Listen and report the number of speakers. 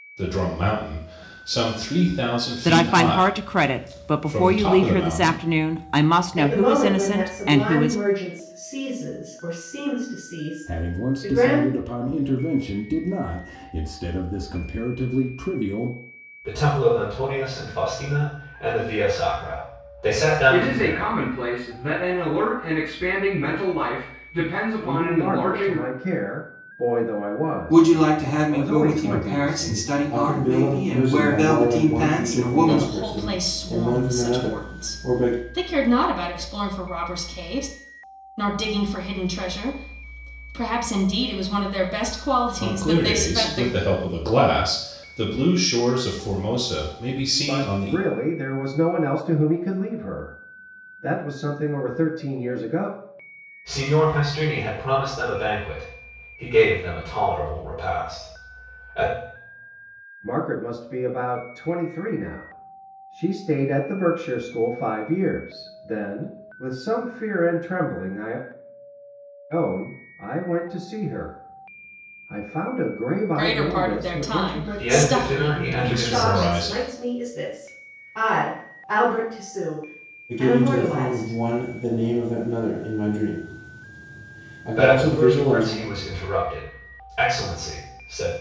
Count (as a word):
ten